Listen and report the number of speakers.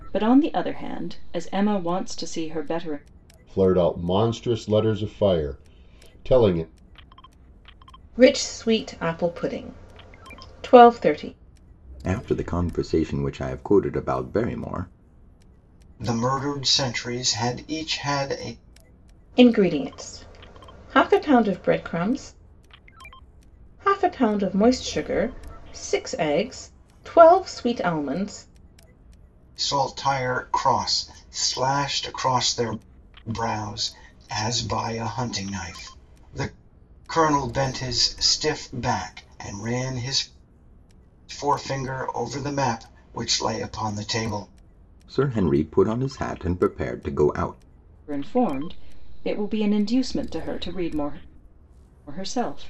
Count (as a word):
five